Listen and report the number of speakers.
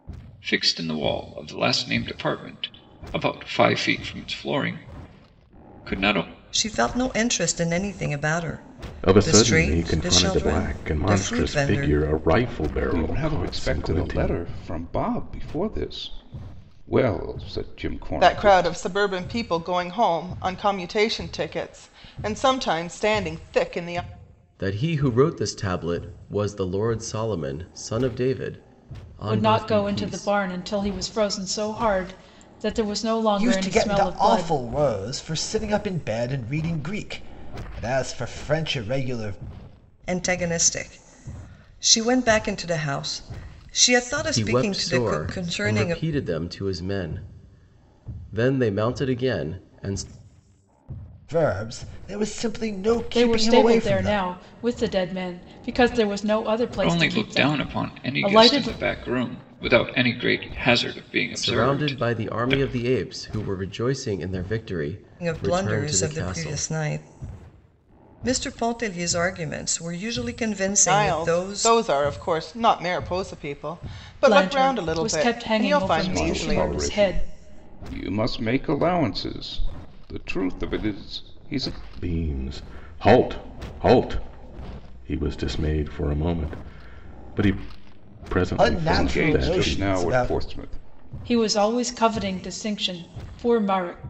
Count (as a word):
eight